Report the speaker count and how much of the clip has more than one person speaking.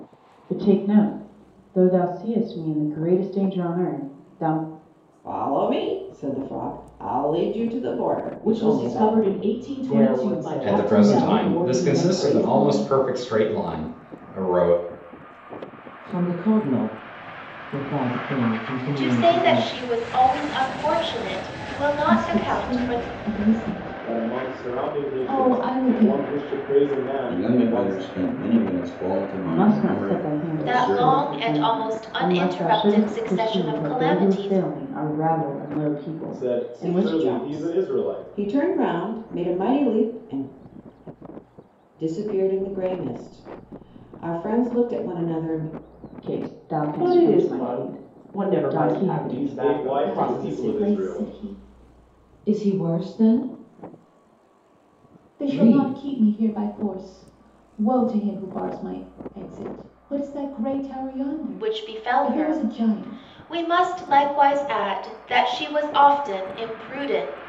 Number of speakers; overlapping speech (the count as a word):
ten, about 35%